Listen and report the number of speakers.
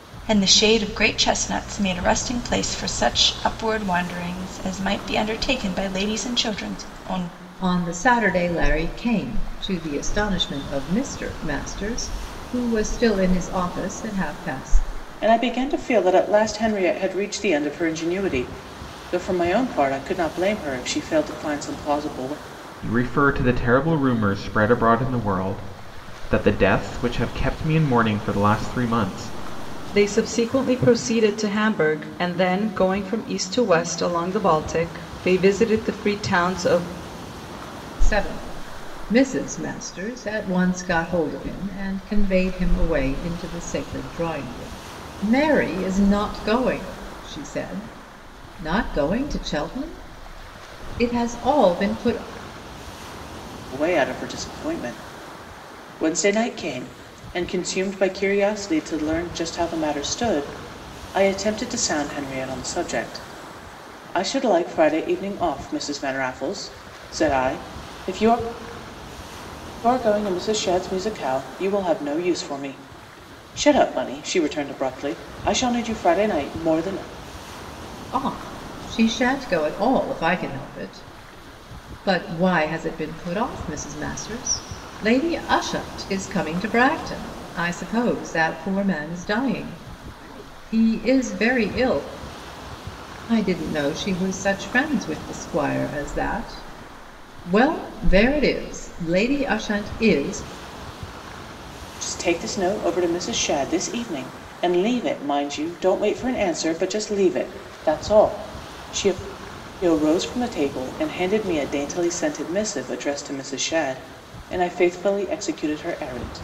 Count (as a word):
five